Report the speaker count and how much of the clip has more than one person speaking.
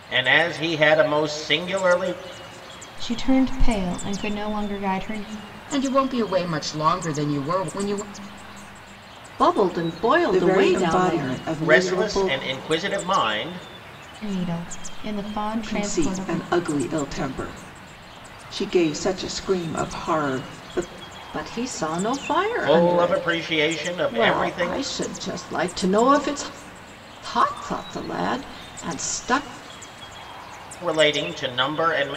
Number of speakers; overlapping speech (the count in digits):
5, about 14%